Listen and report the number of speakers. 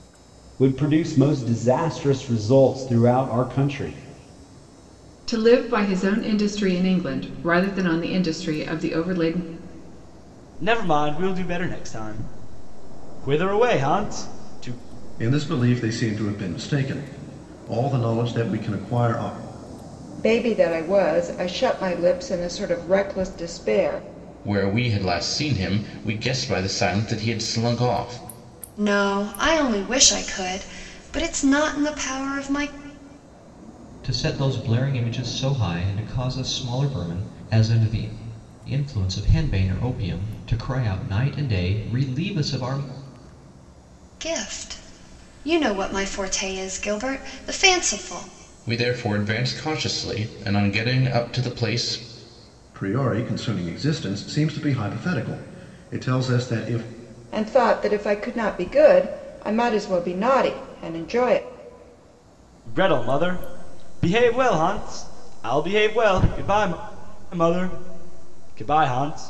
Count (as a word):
eight